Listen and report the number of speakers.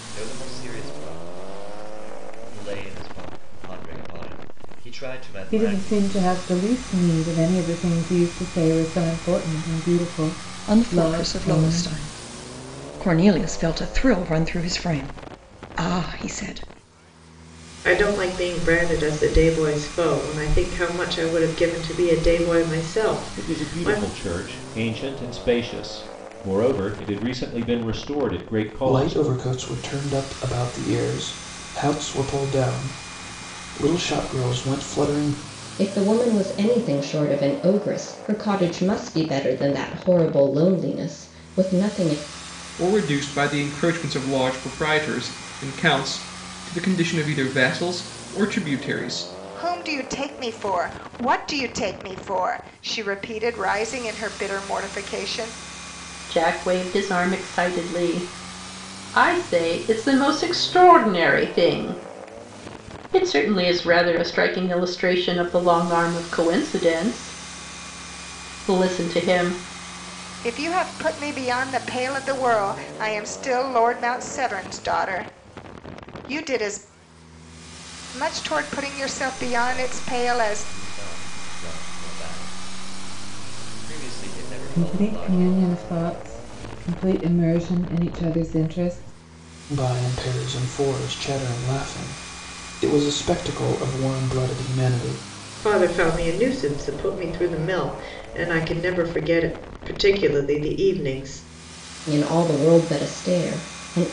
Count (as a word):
ten